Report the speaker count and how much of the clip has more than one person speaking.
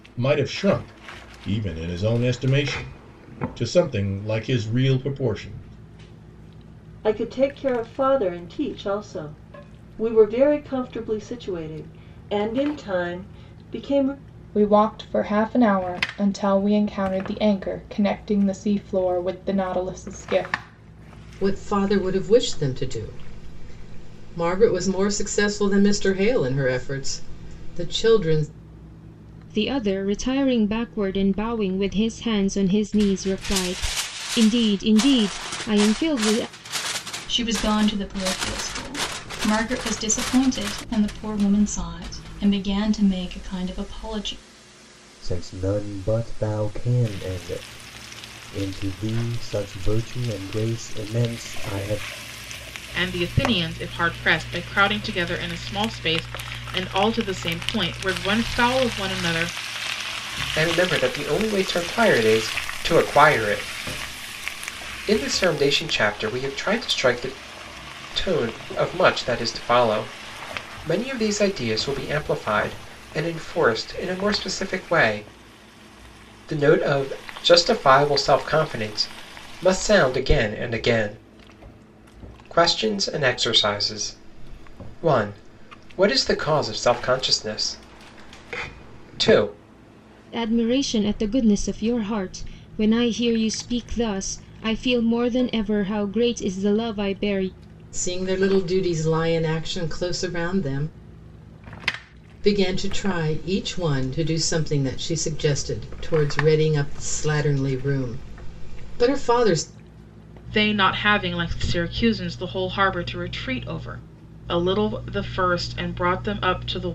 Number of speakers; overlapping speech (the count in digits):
9, no overlap